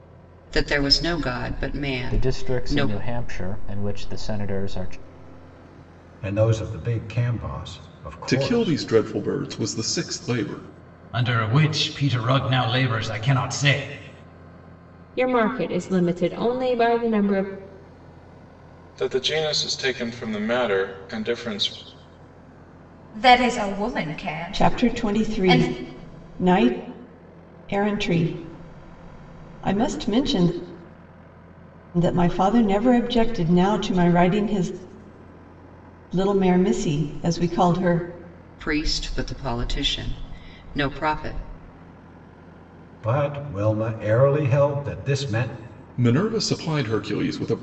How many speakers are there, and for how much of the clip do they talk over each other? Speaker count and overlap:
9, about 6%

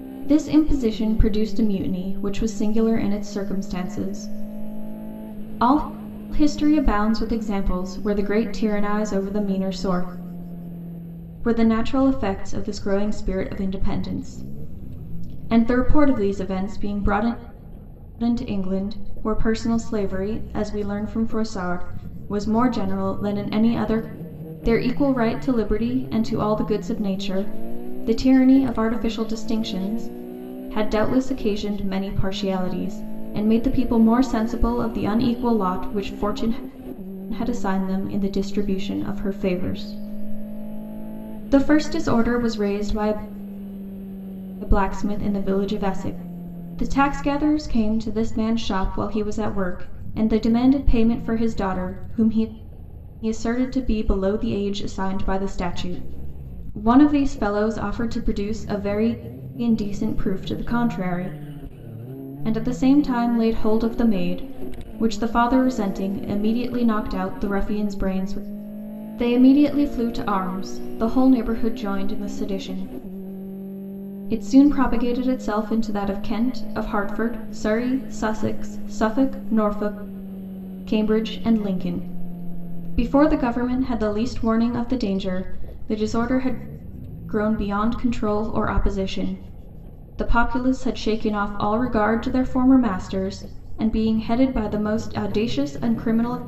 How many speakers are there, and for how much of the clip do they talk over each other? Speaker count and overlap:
1, no overlap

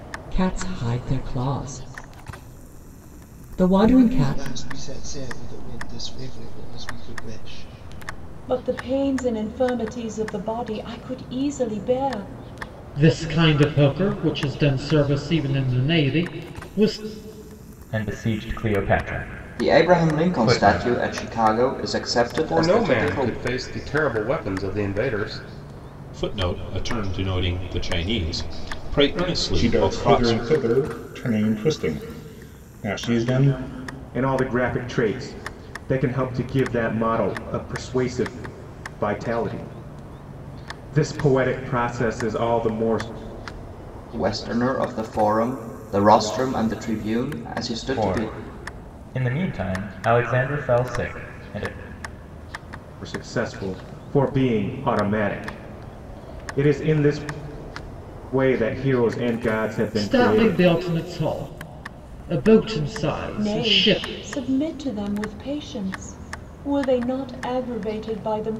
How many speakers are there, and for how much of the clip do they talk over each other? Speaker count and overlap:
10, about 8%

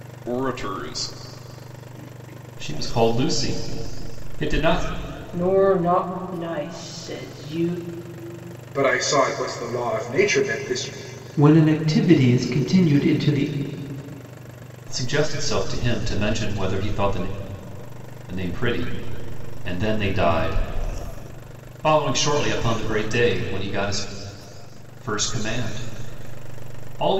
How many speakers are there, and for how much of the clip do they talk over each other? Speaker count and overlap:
5, no overlap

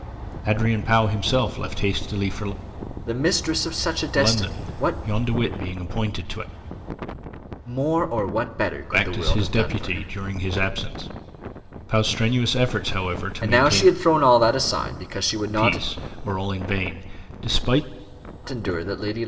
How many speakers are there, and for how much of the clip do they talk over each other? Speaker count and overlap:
2, about 16%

